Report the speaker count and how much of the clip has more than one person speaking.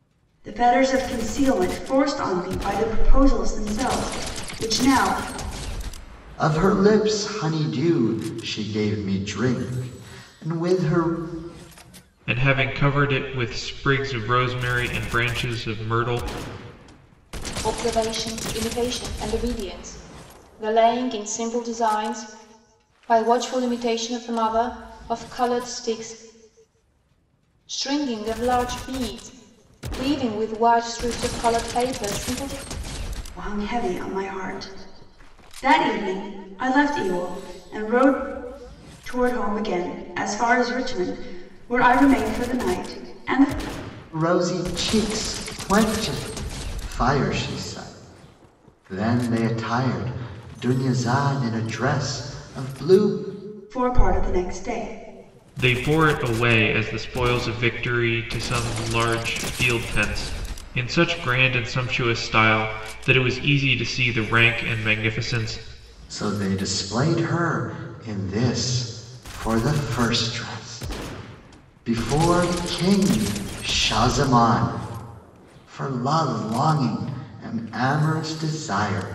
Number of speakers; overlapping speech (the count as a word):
four, no overlap